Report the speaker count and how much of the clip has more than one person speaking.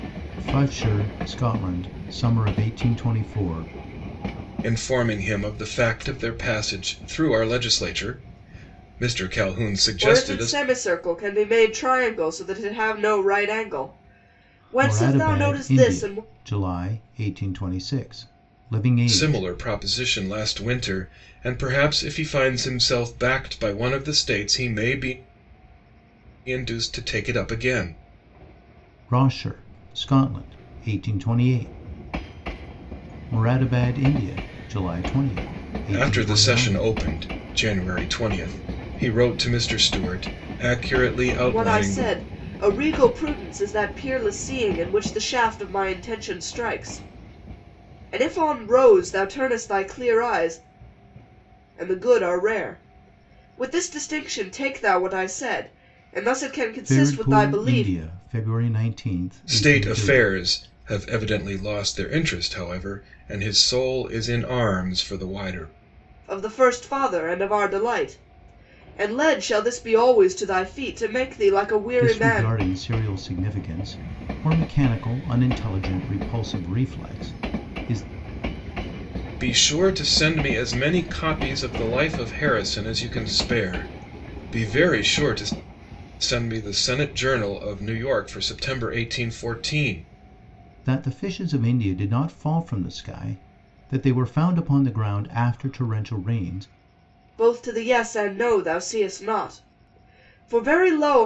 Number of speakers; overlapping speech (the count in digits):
3, about 7%